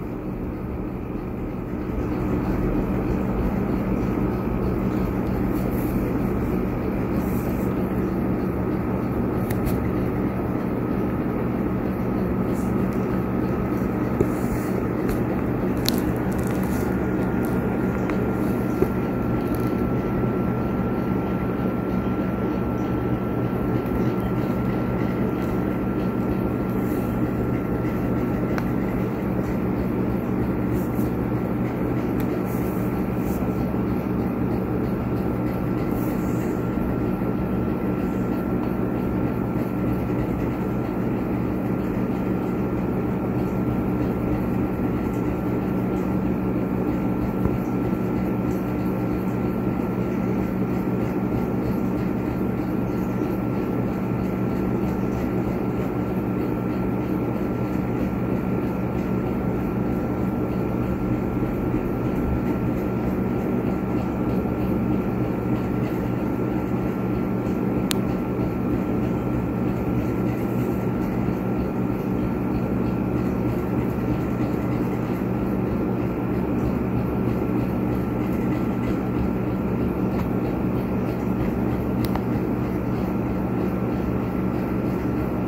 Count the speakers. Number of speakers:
0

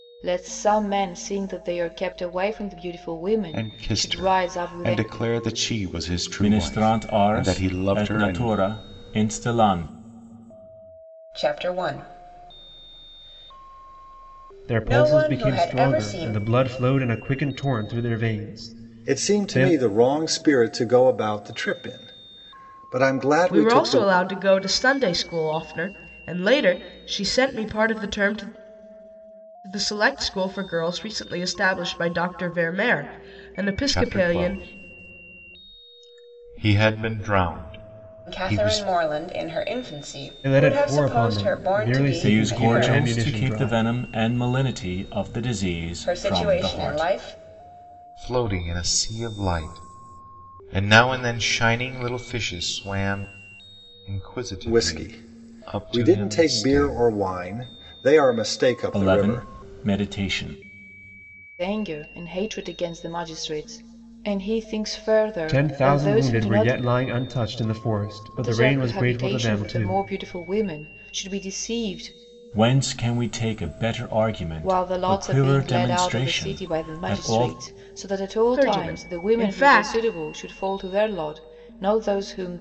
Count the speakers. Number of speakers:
7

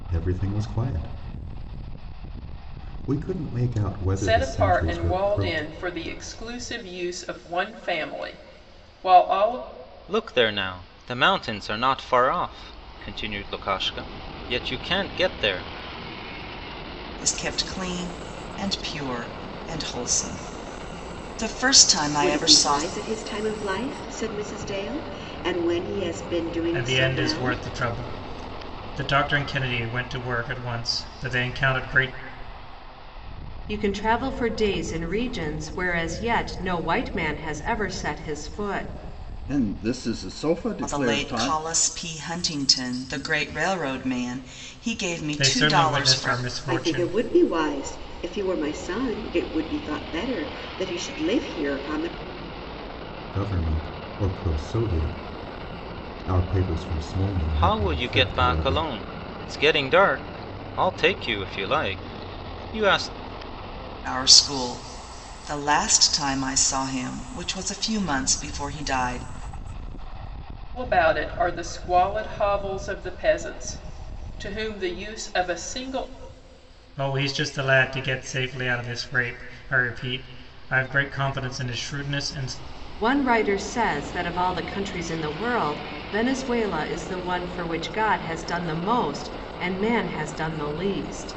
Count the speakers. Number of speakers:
8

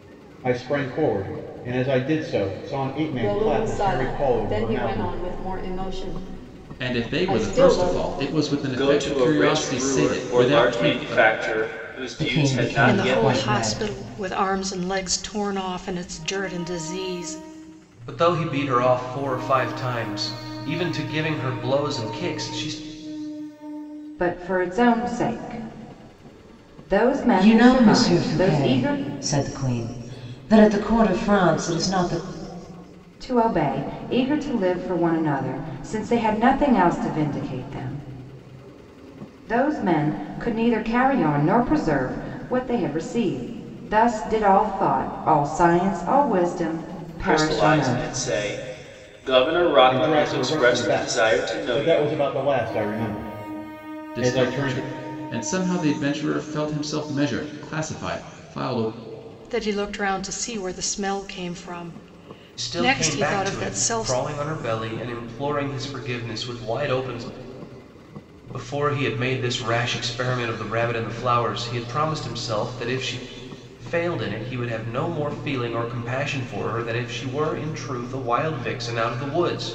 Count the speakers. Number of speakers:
8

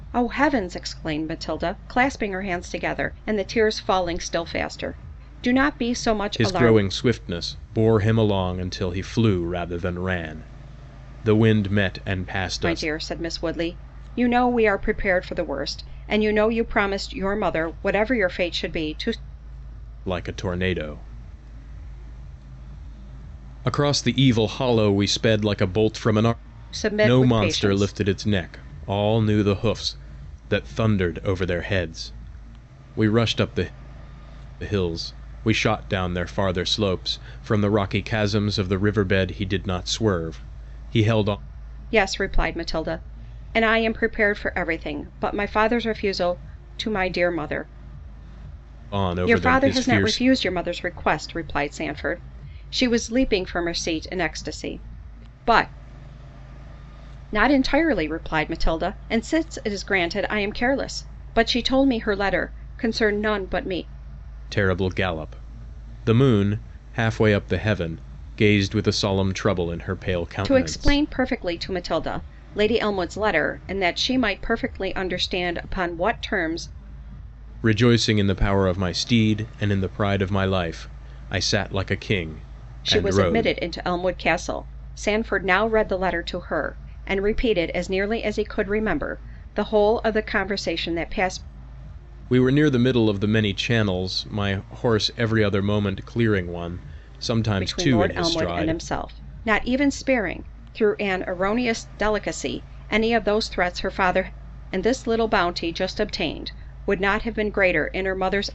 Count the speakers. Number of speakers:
2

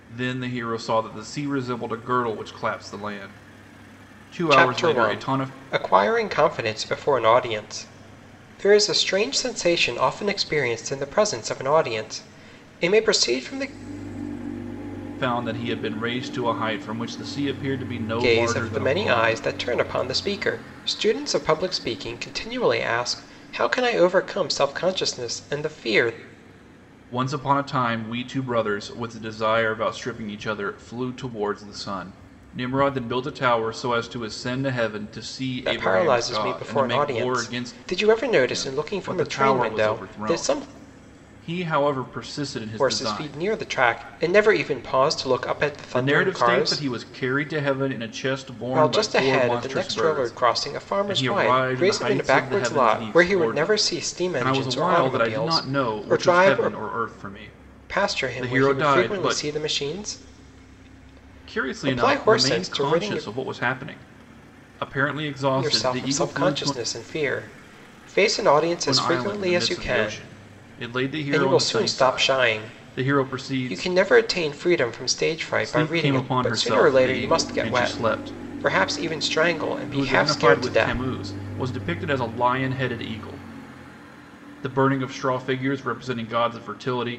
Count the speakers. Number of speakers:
2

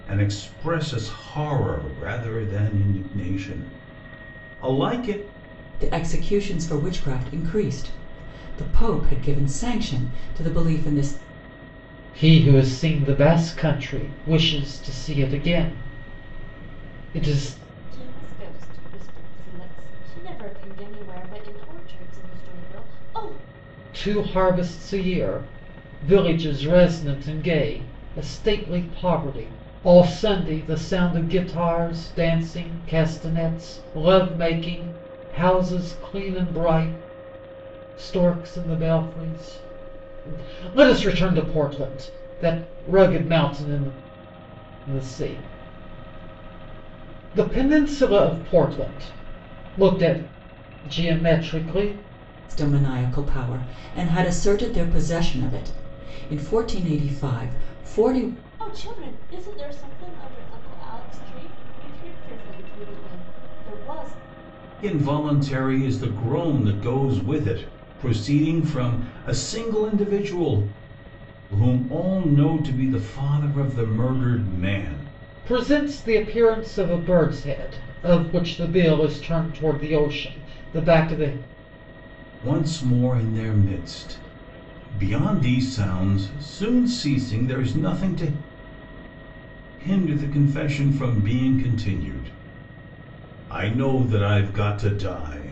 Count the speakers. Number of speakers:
4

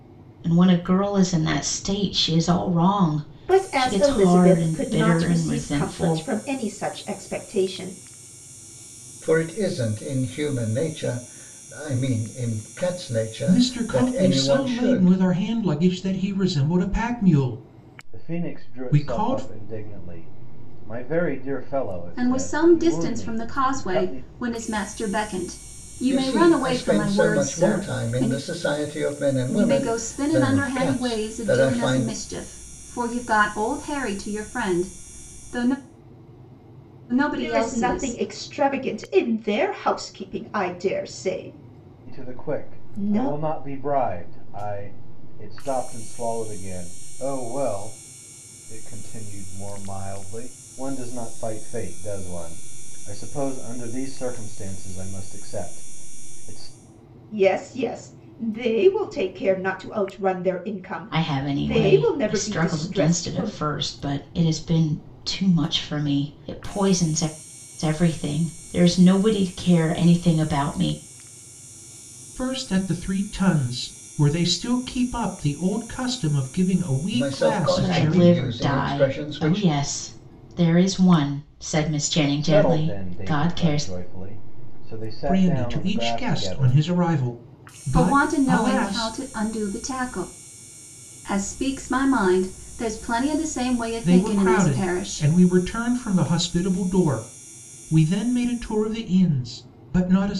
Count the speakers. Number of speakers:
6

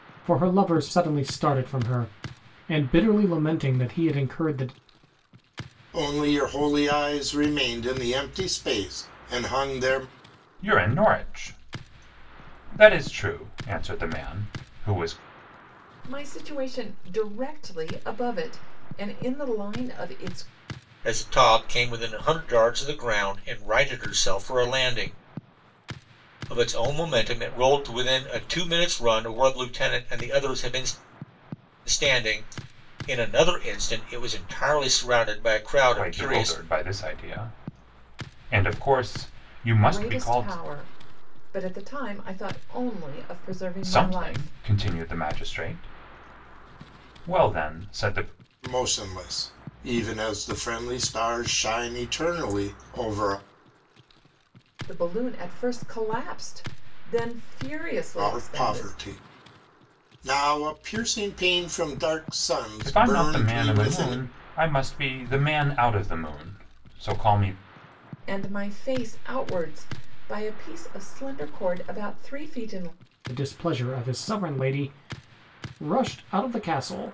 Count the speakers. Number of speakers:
5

